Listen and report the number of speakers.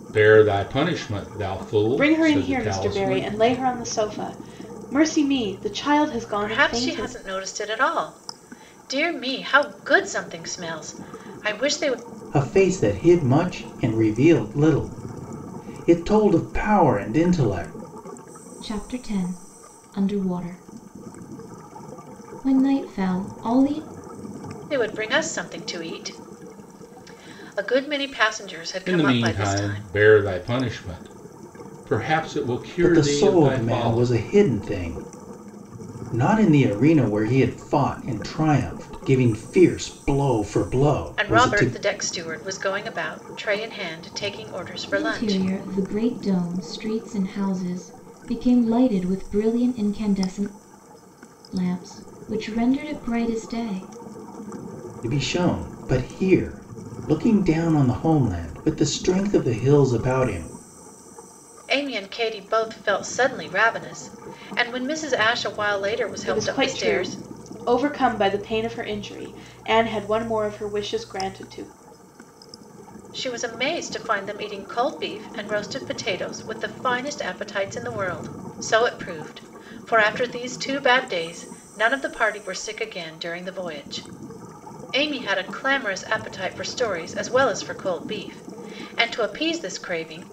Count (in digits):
5